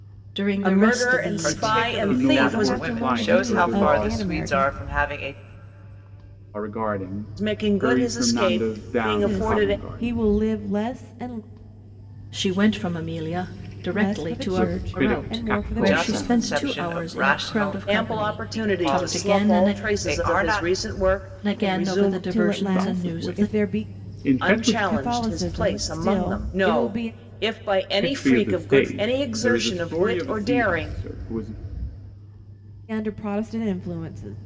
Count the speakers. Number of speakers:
5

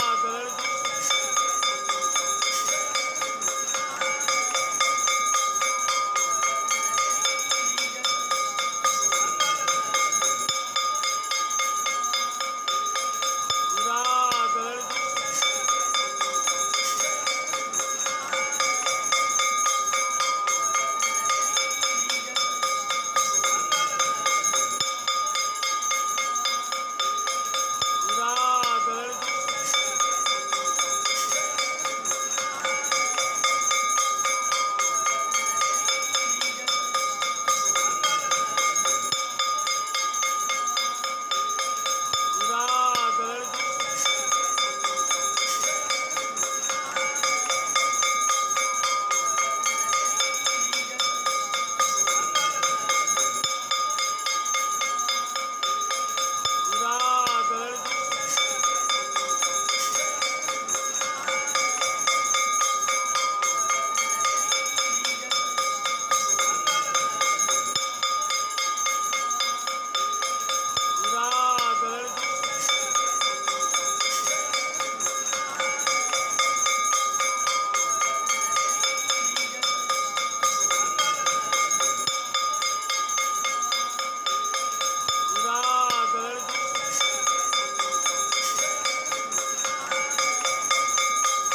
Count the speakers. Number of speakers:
0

